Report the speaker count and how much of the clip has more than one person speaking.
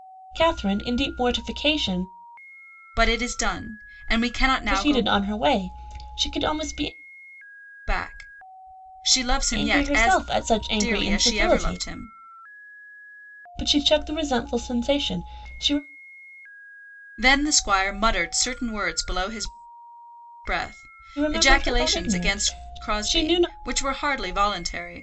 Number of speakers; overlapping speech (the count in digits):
2, about 18%